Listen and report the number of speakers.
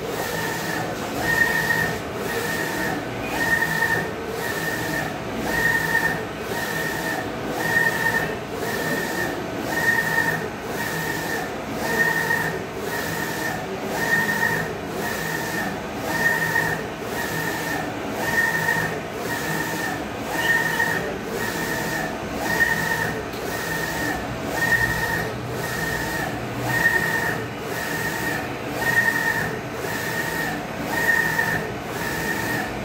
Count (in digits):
0